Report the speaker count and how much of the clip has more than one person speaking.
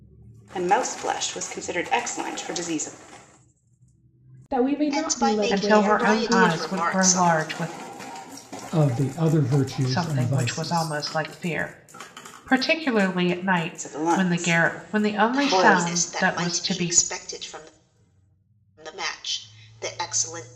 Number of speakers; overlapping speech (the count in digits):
5, about 33%